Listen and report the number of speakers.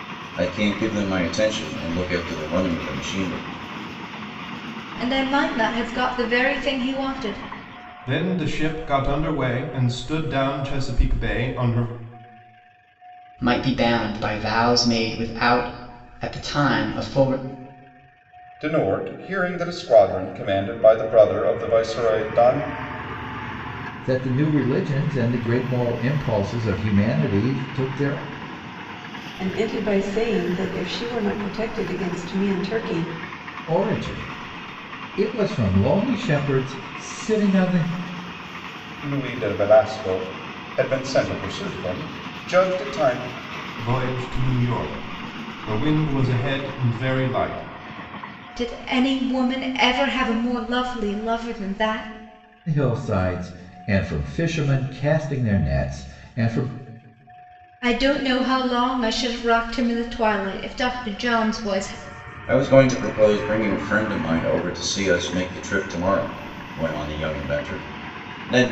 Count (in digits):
7